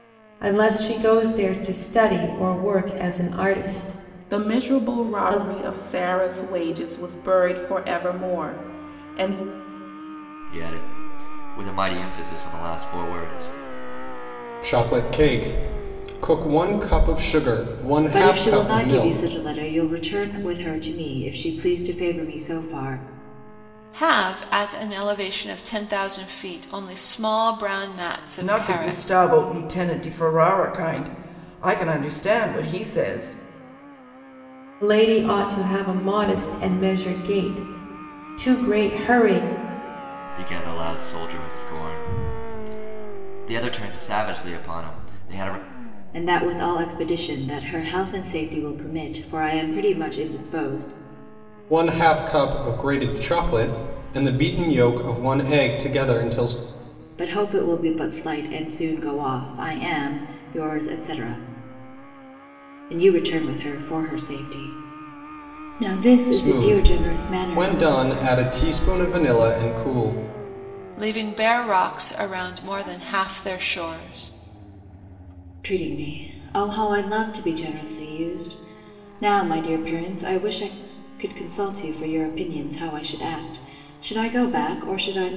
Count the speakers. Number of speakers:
7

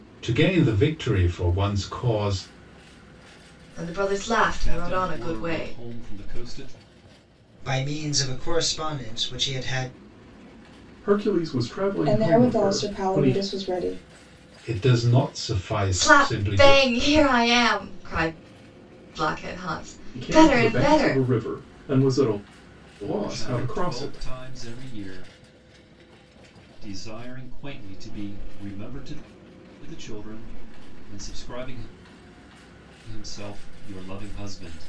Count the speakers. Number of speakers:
6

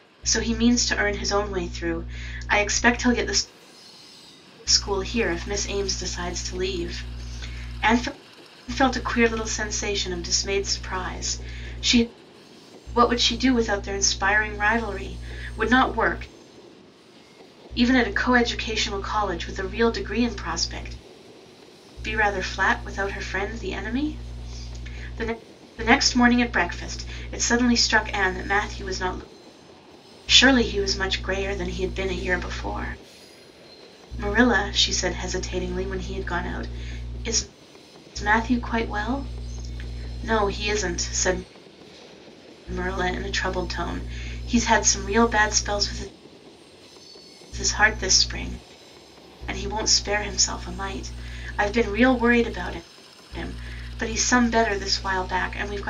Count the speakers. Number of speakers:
1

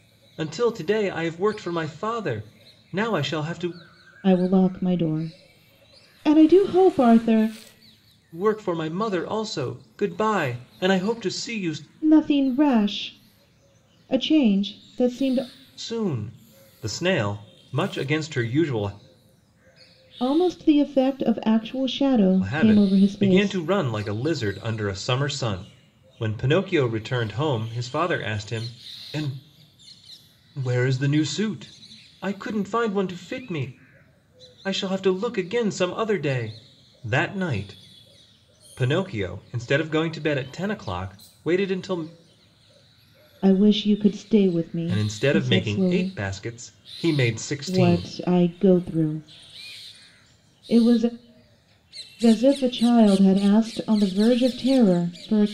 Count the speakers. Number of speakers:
2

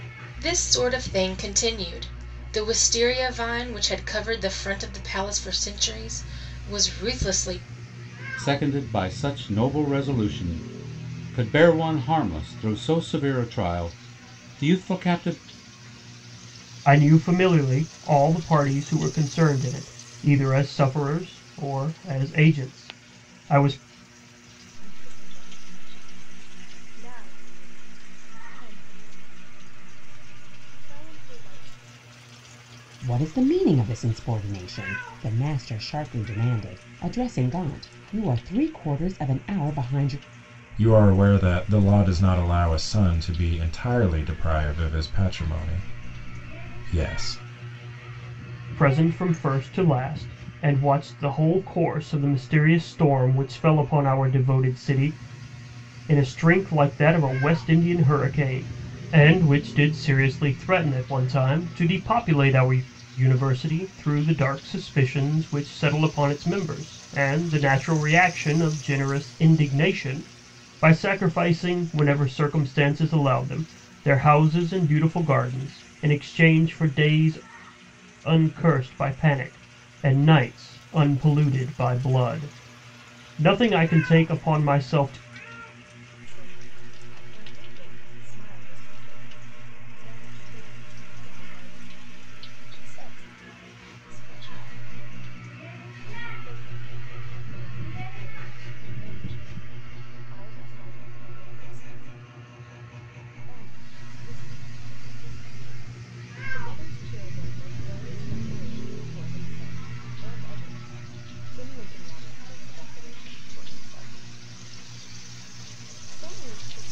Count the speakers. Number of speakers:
6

